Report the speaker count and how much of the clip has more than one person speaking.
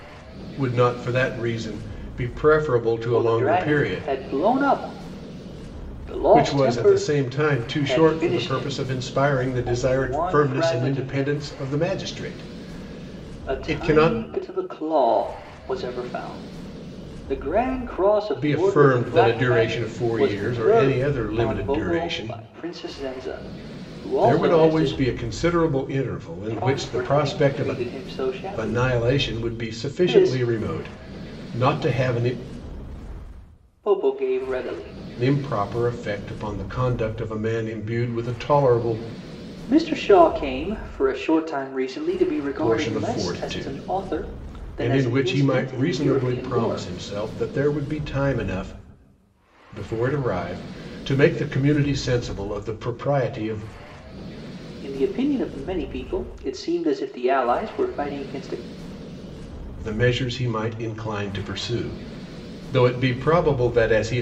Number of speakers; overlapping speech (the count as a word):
two, about 27%